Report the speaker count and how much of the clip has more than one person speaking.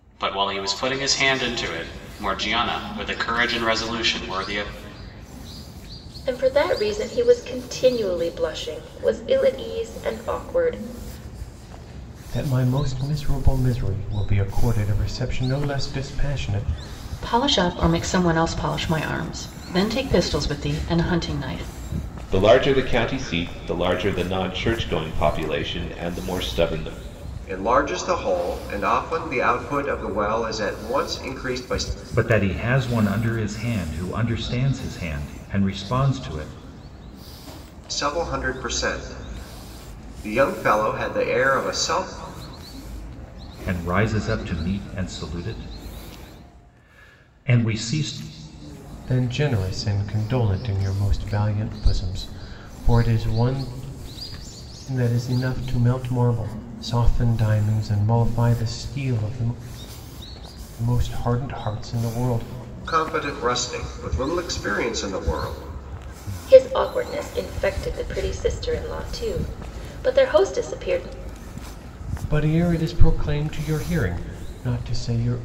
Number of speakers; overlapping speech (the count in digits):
7, no overlap